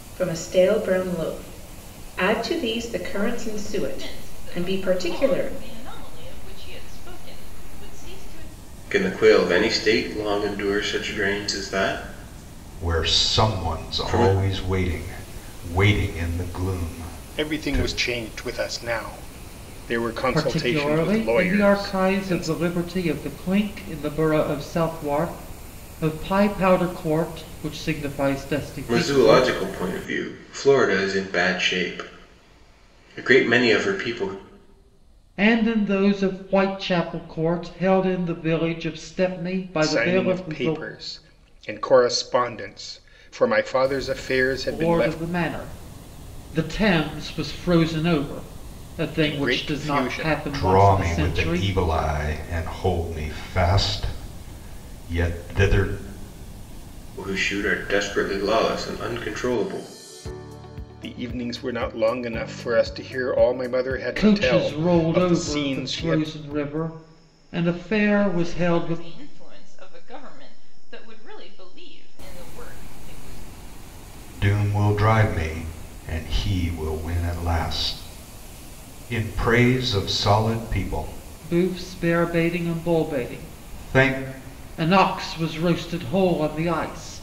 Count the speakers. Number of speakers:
6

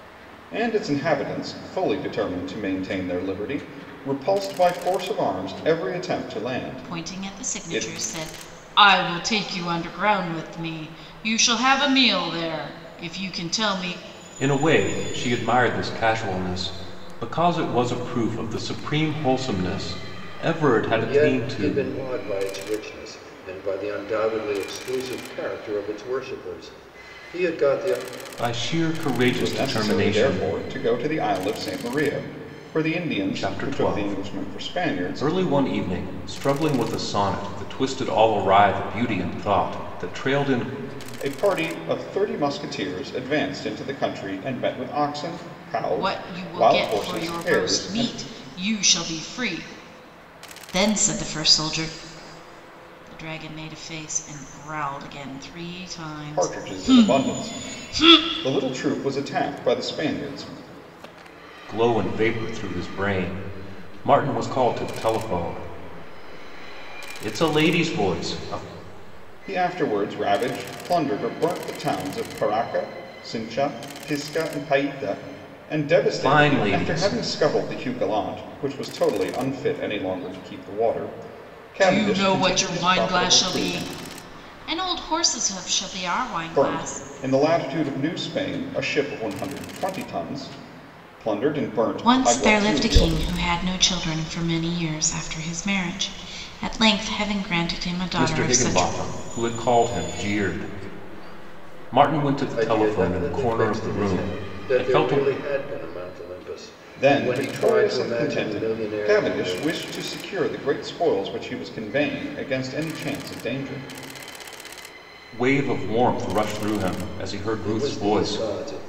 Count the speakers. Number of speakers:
4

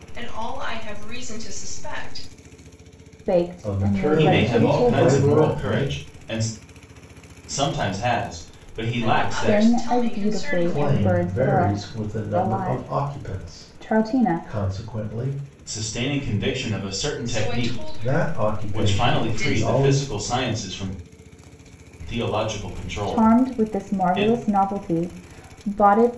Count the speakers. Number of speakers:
4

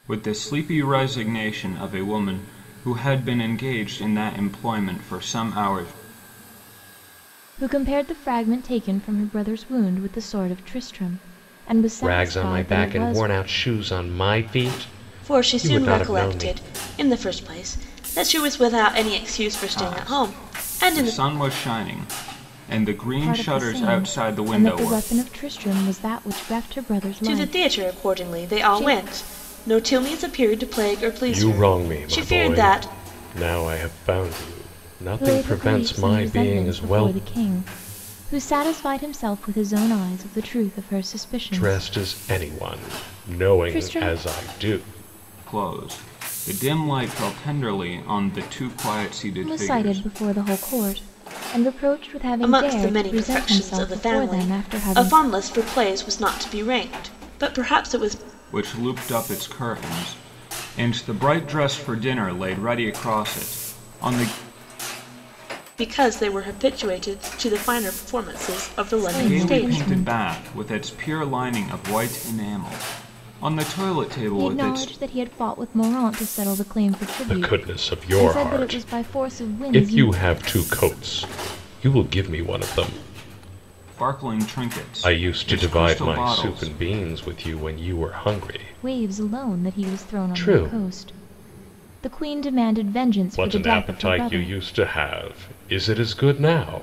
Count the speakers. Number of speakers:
4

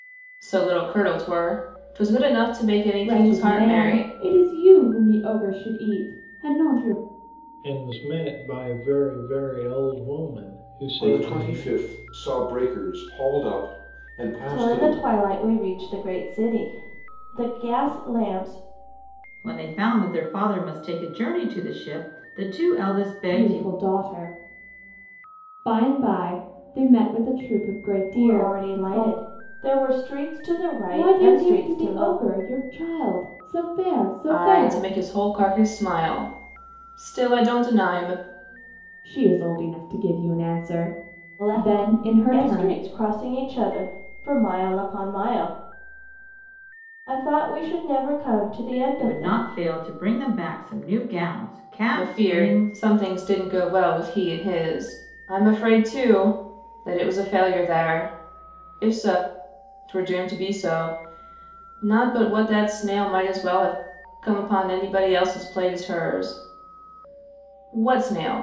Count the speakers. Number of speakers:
6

